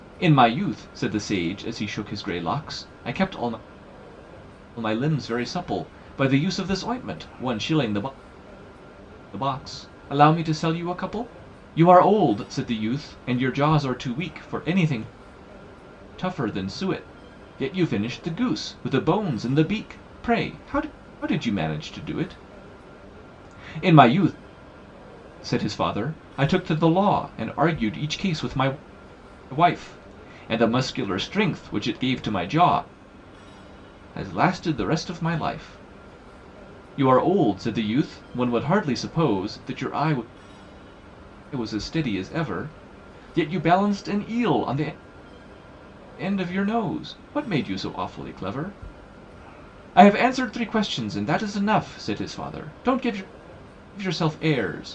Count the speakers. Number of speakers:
1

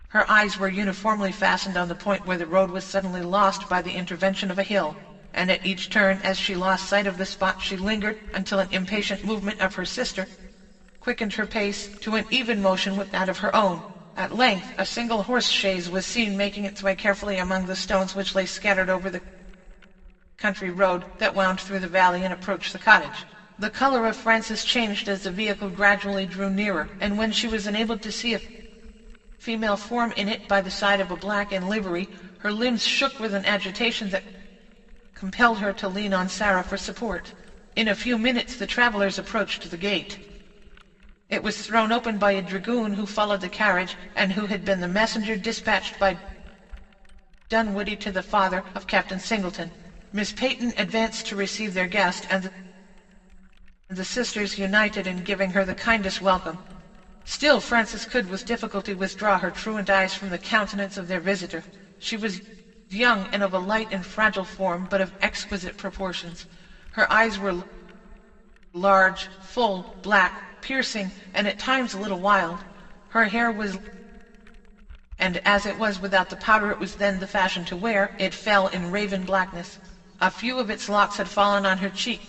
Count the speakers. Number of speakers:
1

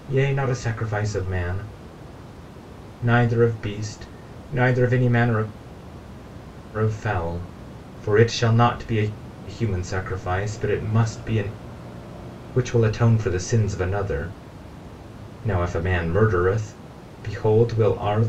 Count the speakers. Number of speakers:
1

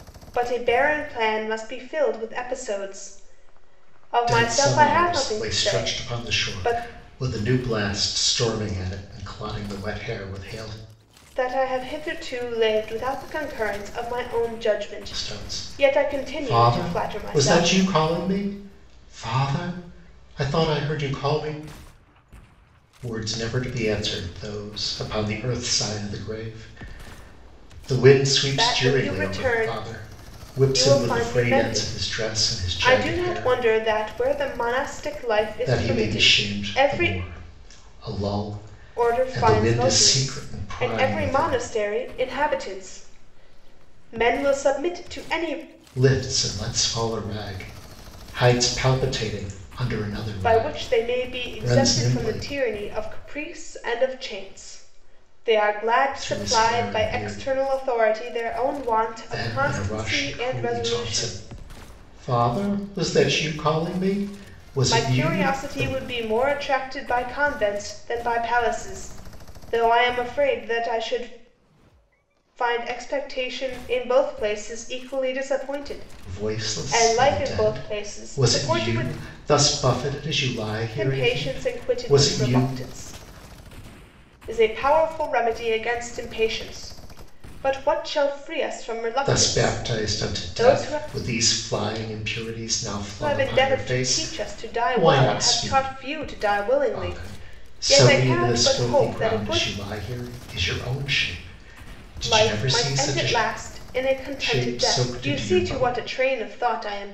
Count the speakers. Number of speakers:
2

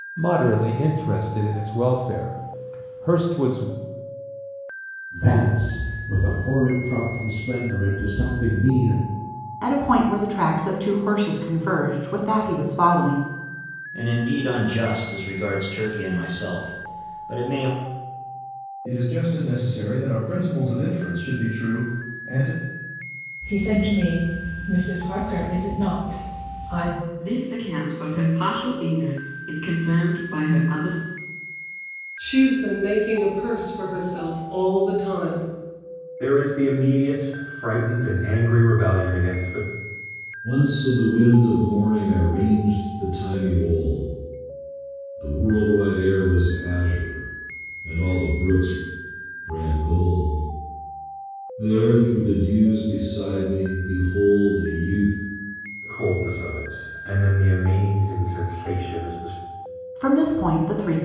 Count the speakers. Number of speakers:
10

